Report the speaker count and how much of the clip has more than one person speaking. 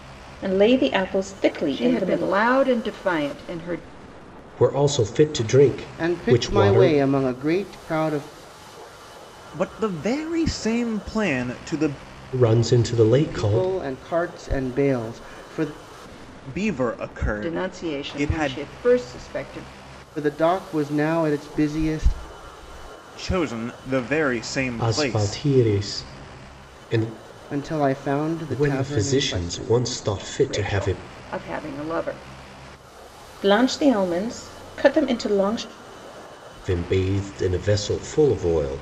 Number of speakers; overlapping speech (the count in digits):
5, about 15%